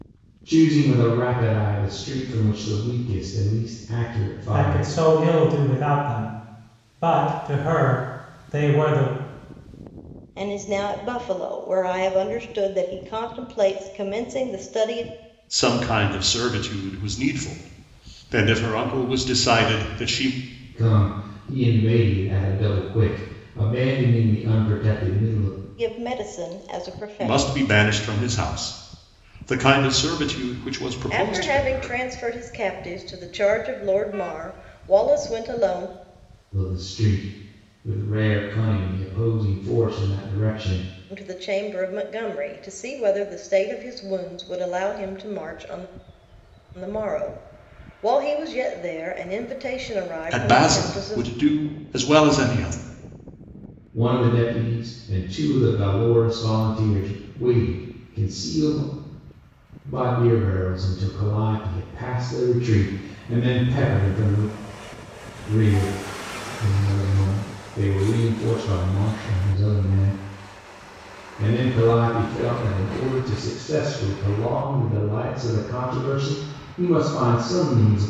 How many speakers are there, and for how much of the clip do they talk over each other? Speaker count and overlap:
four, about 4%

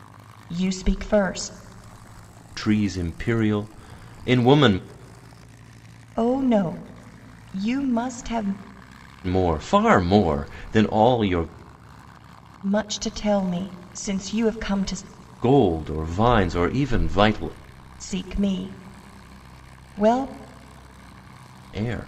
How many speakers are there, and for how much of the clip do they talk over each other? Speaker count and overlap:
two, no overlap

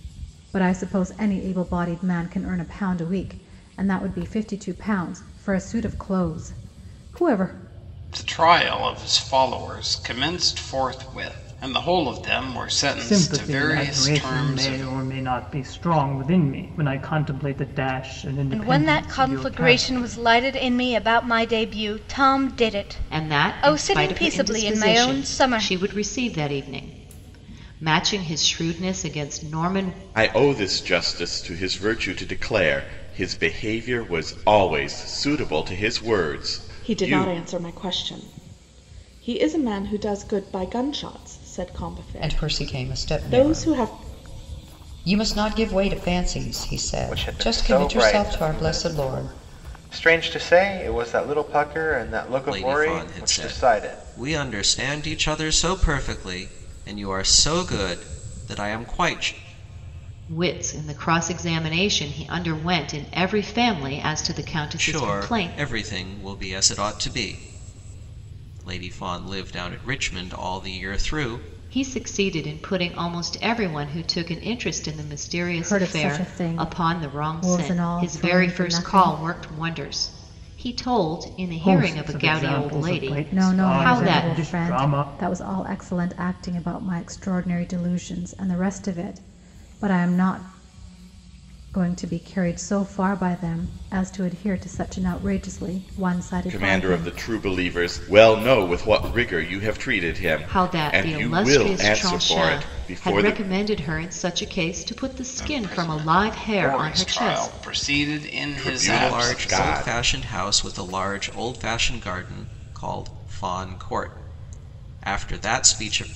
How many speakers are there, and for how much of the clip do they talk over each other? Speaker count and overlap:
ten, about 24%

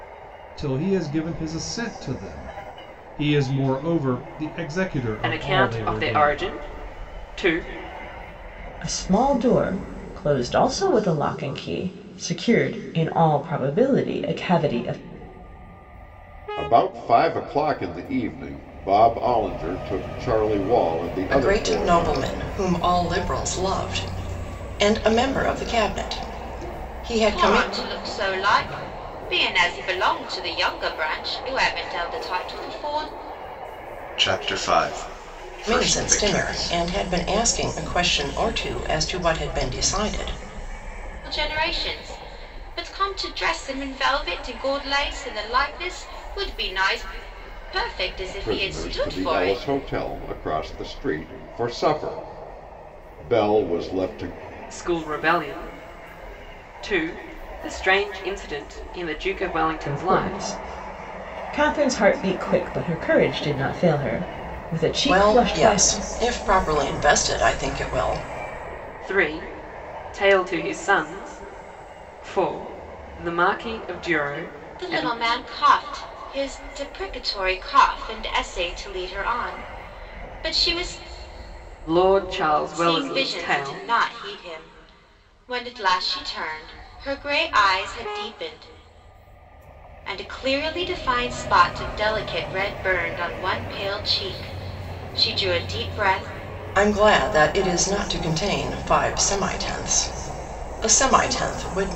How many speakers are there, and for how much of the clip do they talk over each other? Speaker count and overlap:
seven, about 8%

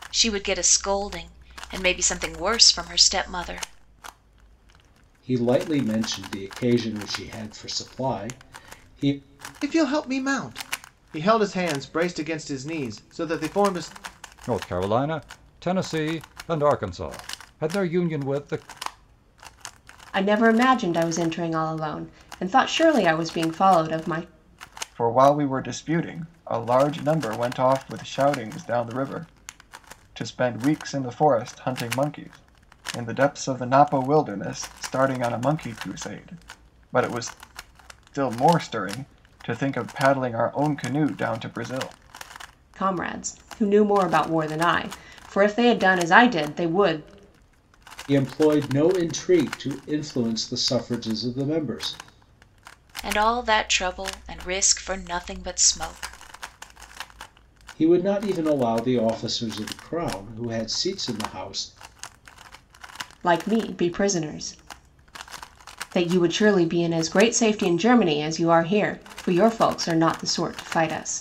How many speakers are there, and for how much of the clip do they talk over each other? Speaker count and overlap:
six, no overlap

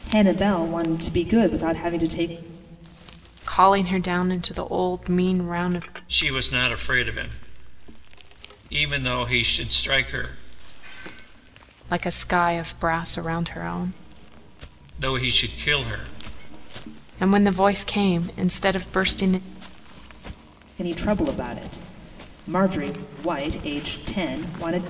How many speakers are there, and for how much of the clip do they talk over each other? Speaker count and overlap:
three, no overlap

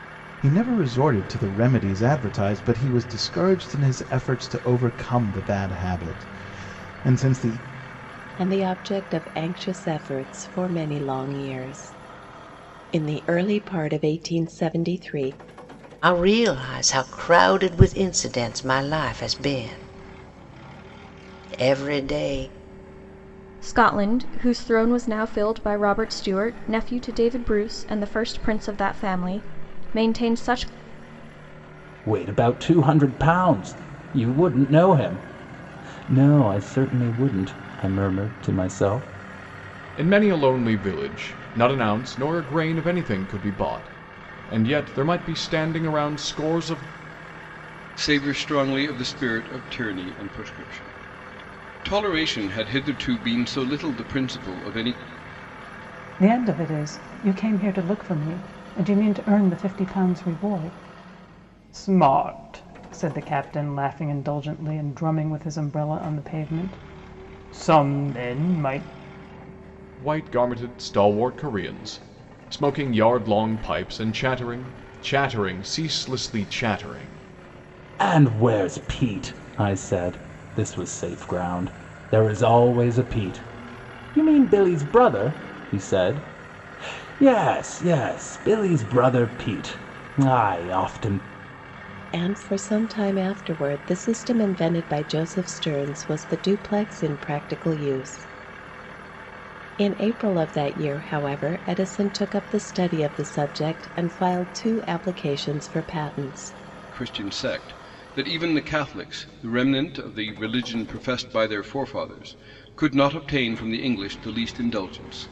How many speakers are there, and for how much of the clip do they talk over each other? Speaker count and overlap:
eight, no overlap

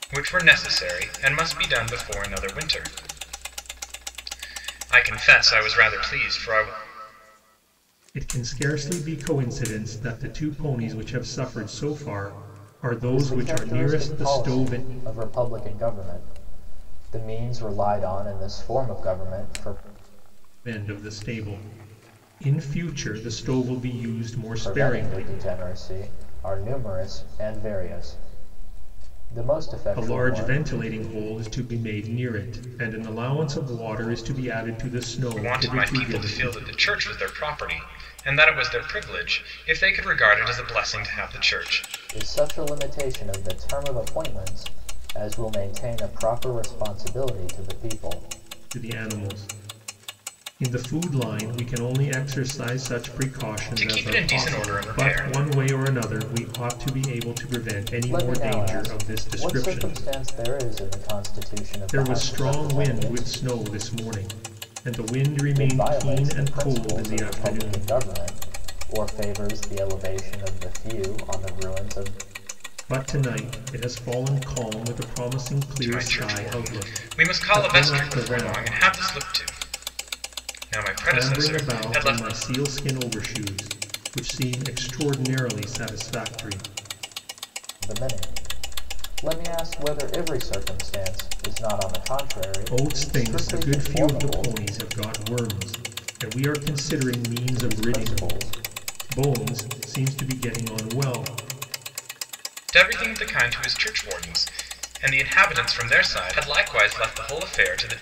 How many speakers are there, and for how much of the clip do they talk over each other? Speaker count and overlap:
three, about 17%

